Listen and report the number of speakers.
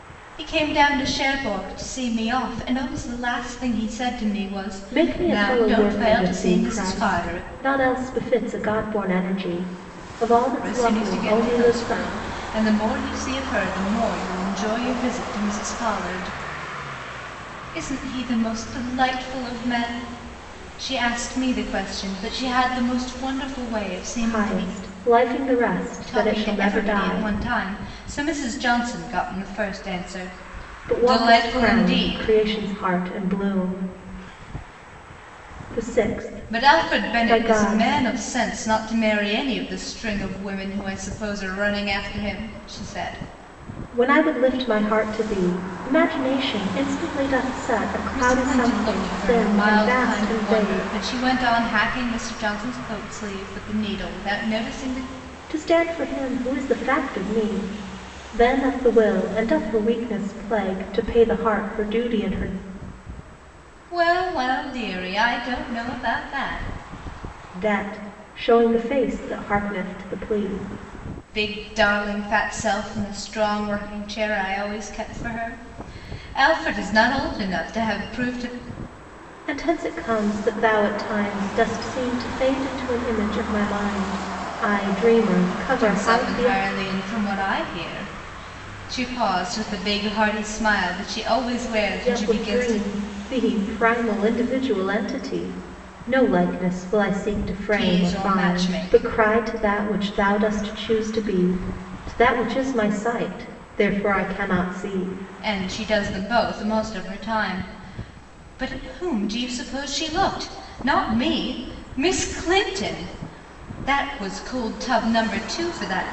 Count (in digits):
2